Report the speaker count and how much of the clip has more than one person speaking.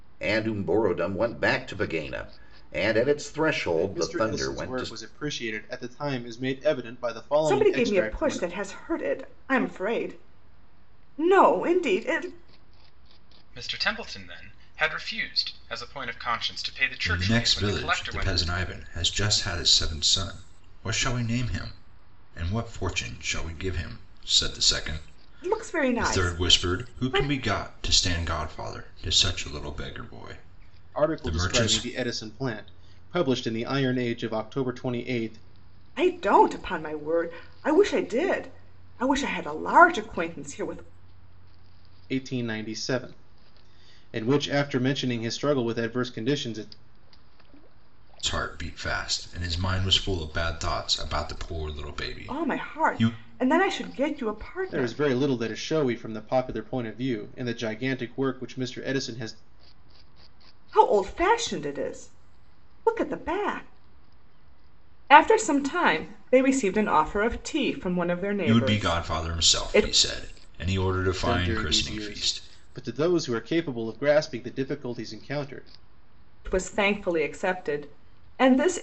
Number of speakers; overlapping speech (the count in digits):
5, about 13%